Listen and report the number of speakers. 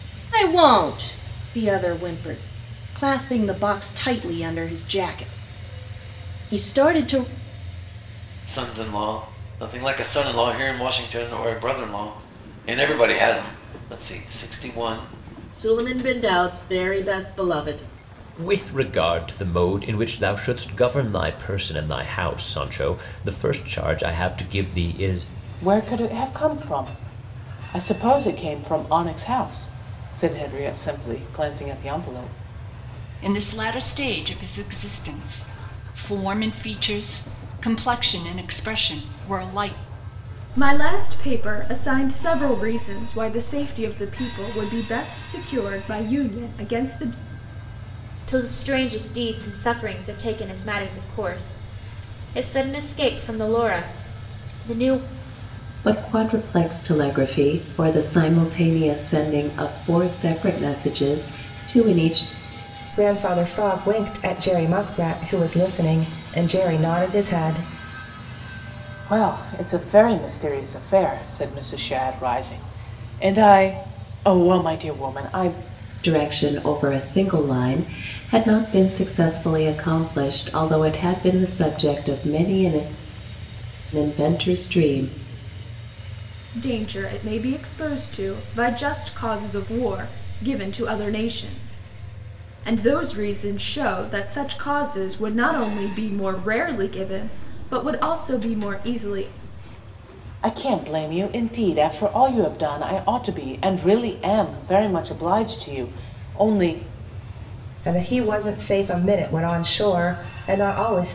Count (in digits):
10